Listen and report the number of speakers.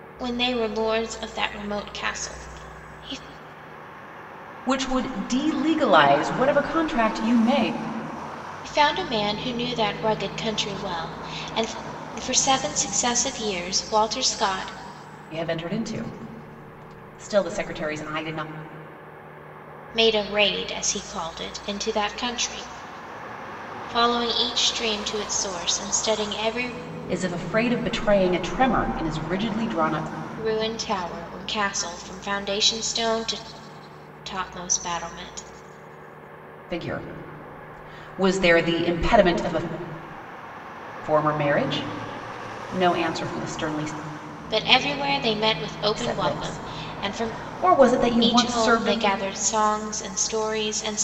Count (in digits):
2